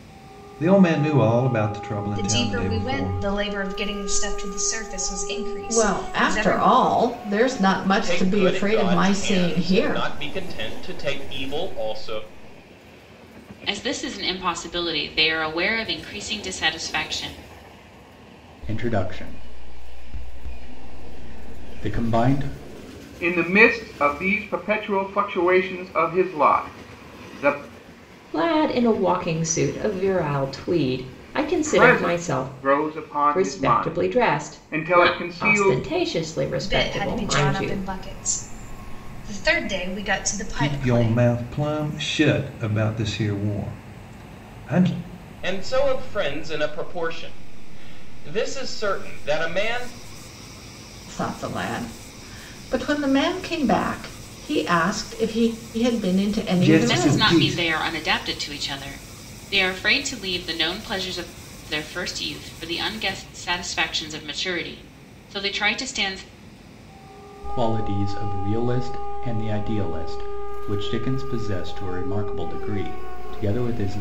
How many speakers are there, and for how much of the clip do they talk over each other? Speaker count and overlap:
8, about 14%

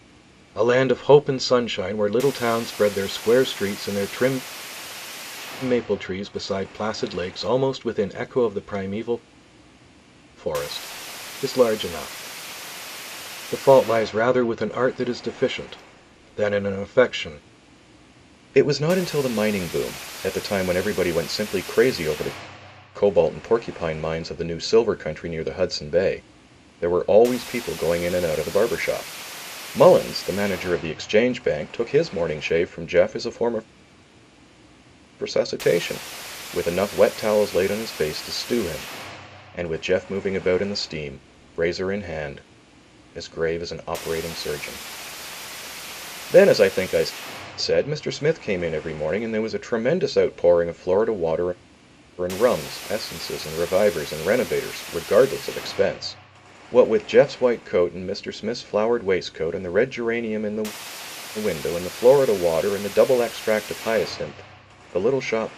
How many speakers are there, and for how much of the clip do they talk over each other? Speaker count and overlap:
1, no overlap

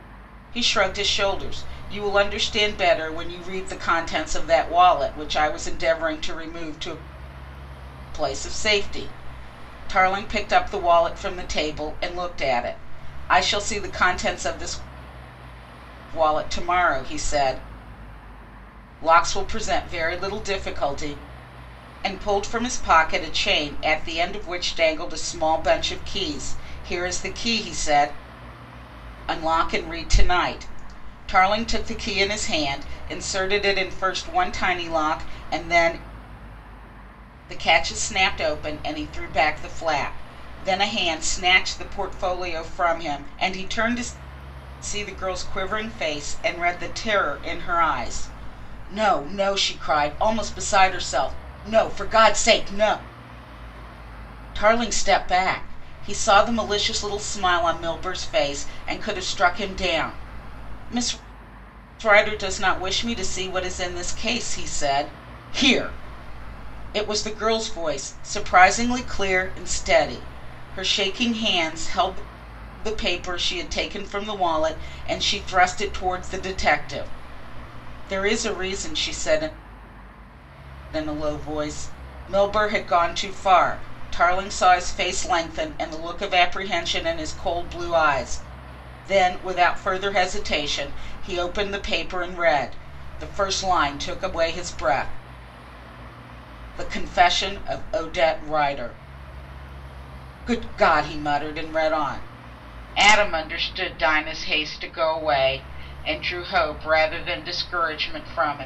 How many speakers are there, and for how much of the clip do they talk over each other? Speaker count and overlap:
1, no overlap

